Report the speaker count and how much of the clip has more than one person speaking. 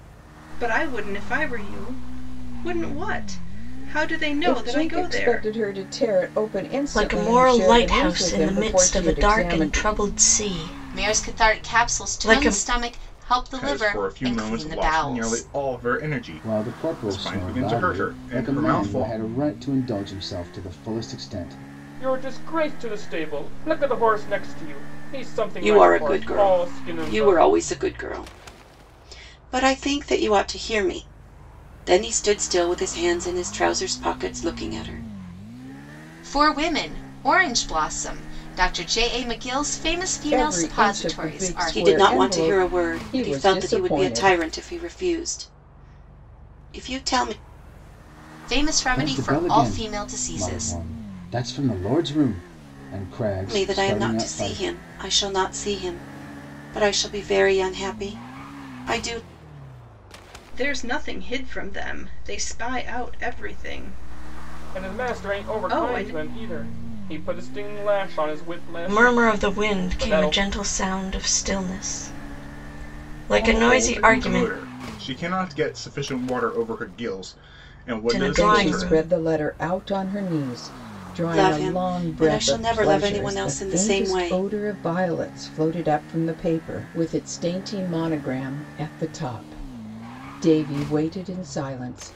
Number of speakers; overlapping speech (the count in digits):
8, about 30%